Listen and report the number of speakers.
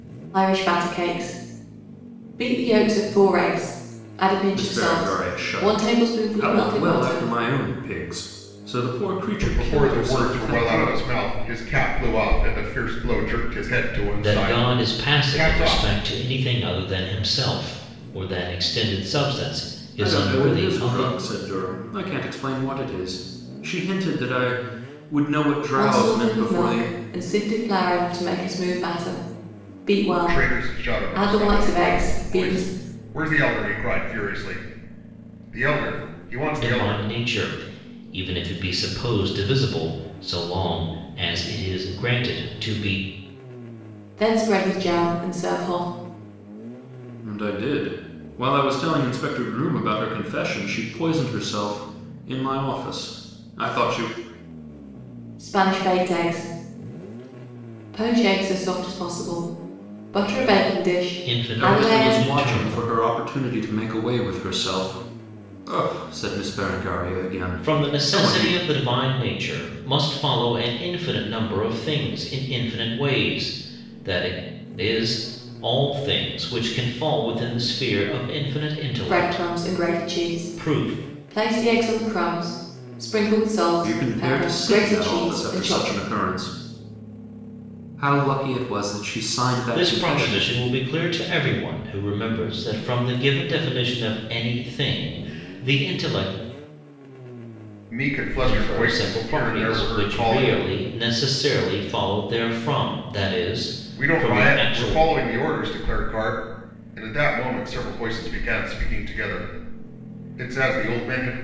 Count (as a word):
four